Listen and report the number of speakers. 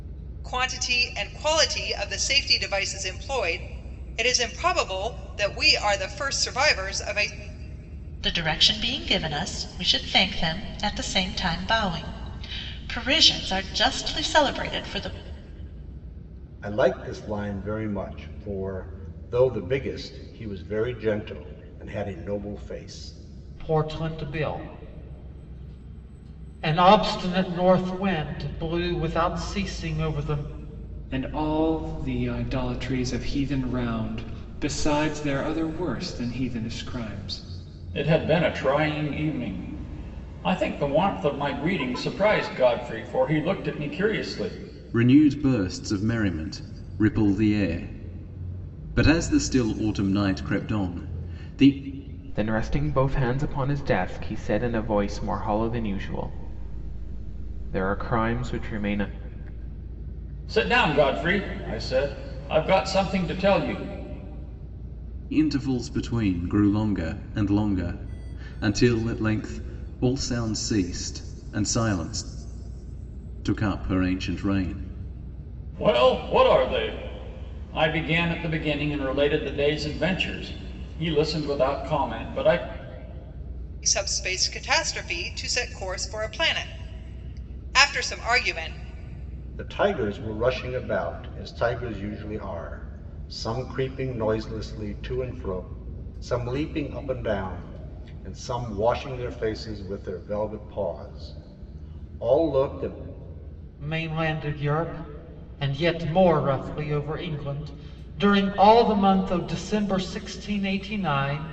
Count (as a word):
eight